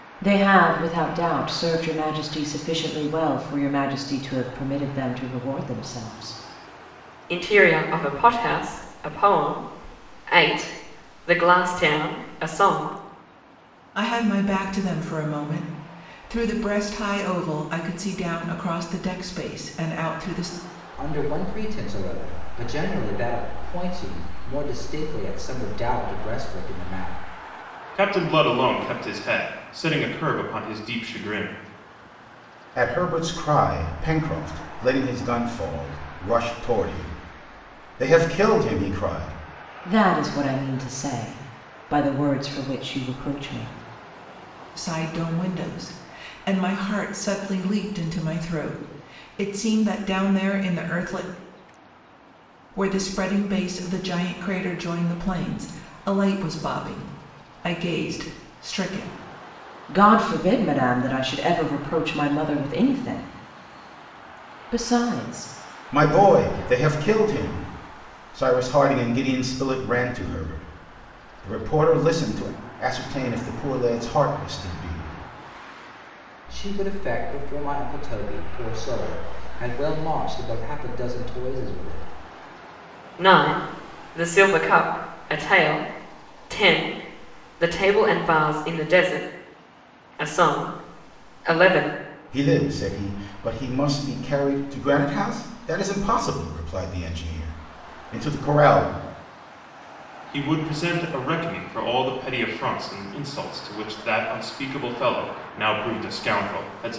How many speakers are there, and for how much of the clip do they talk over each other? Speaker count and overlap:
six, no overlap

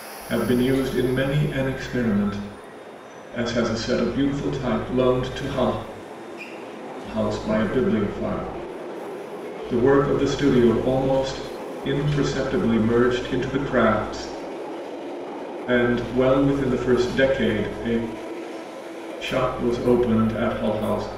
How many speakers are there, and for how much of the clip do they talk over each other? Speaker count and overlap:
one, no overlap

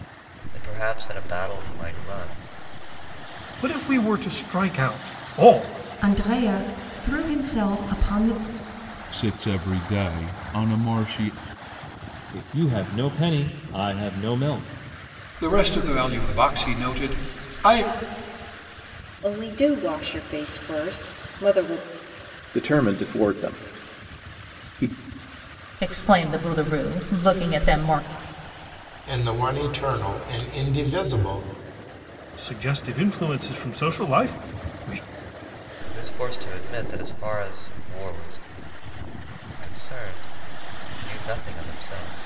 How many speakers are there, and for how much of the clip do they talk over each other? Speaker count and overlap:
ten, no overlap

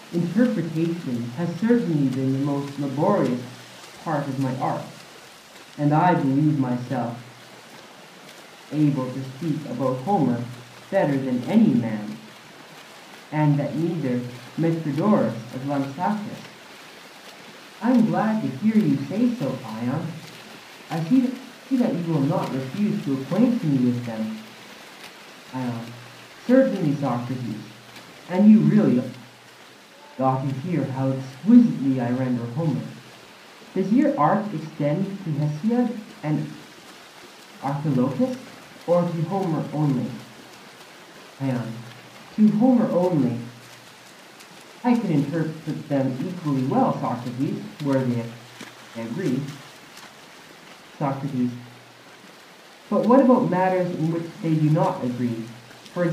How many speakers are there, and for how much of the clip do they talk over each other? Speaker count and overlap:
one, no overlap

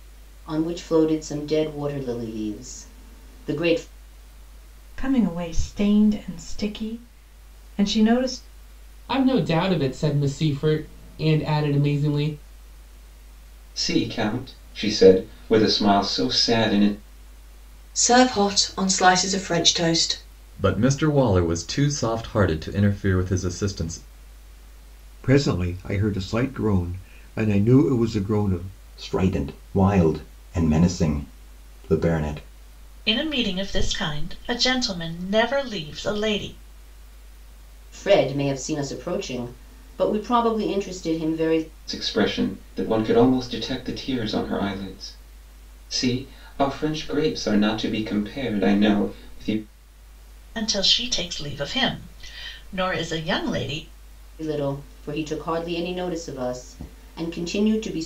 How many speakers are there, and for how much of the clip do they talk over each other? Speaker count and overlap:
nine, no overlap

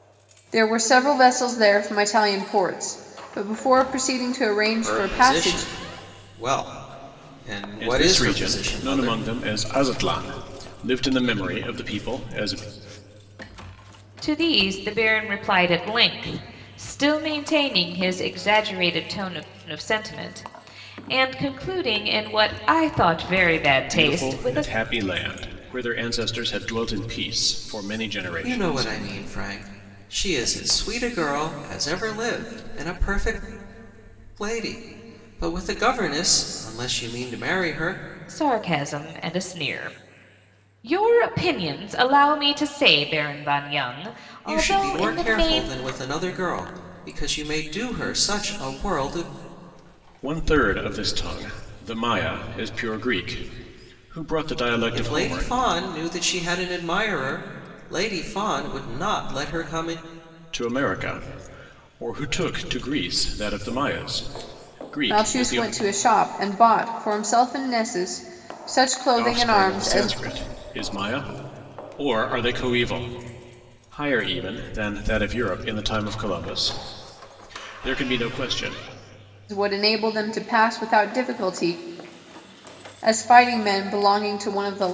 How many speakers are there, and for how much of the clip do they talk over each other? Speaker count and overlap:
four, about 9%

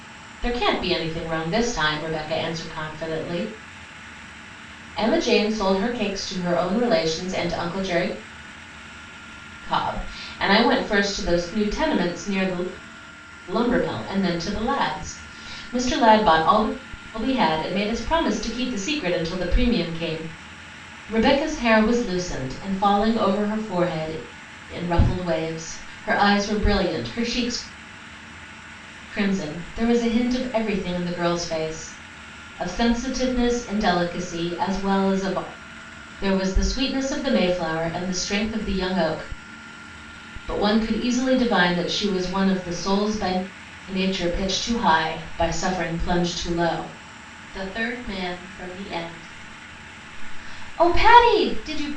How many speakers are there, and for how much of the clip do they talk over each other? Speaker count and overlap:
one, no overlap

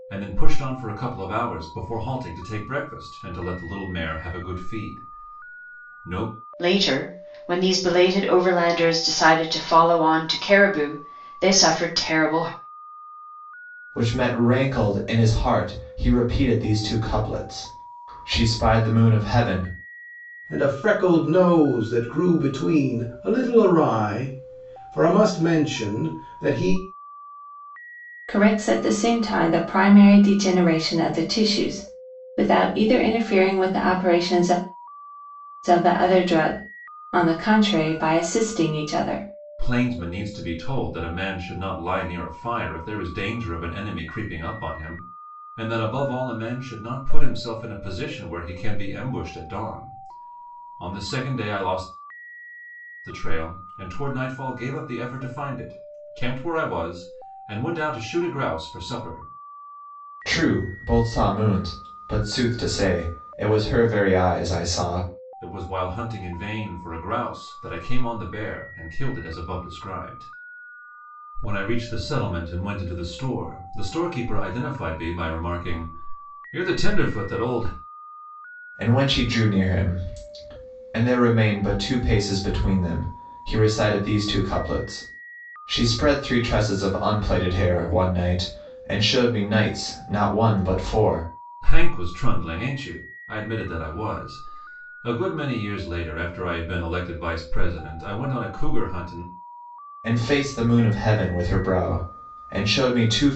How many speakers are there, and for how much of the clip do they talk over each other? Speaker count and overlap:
five, no overlap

